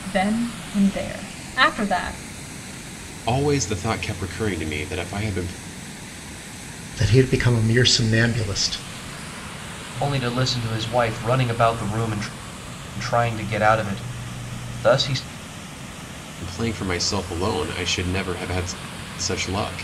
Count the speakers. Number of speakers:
4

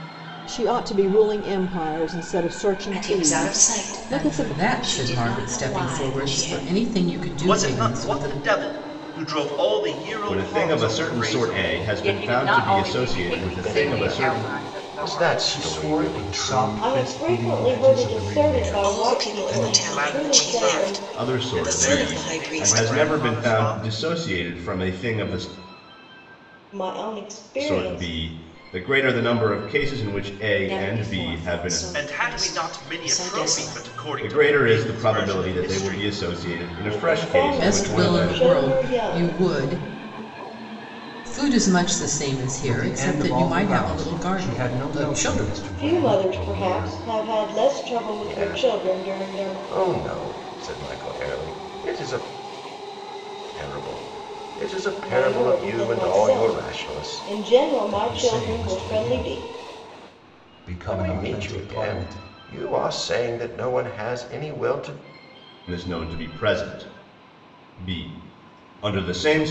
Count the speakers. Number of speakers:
10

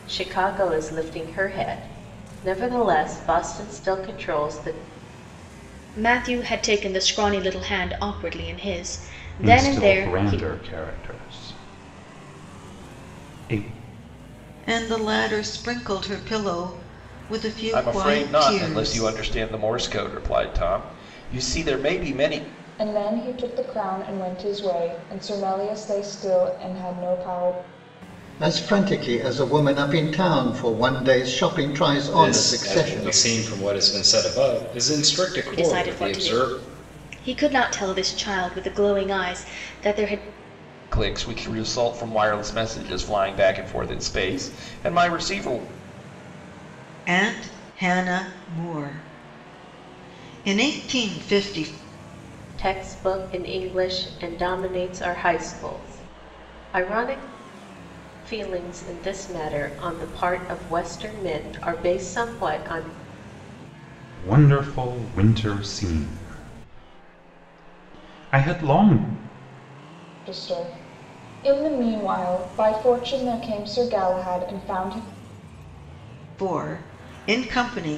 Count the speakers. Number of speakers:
8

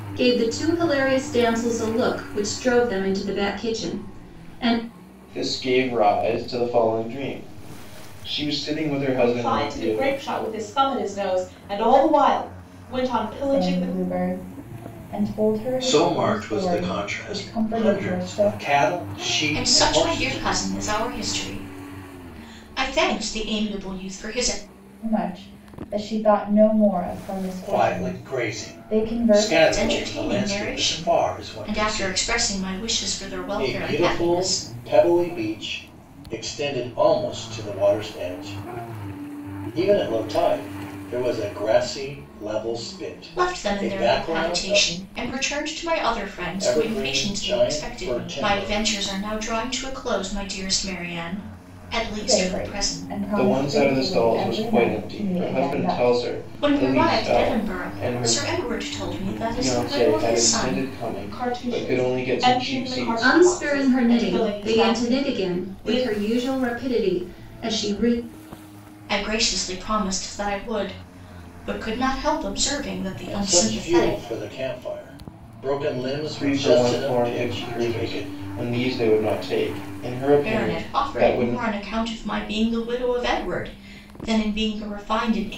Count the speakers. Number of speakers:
6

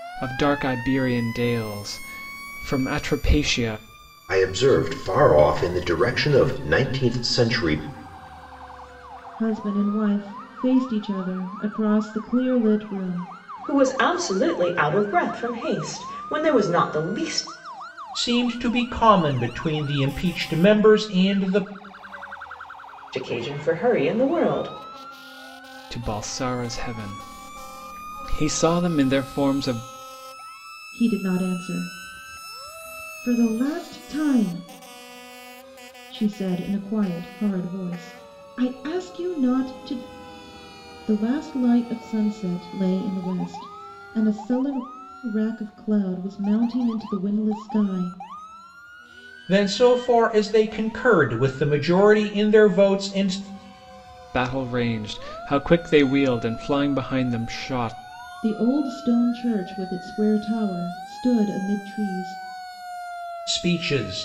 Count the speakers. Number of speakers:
5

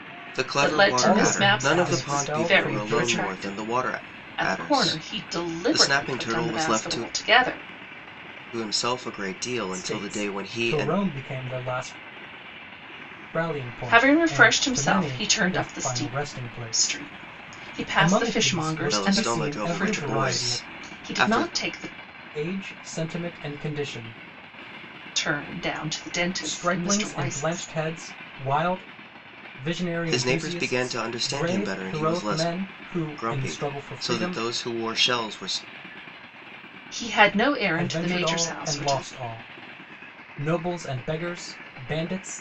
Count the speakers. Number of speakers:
3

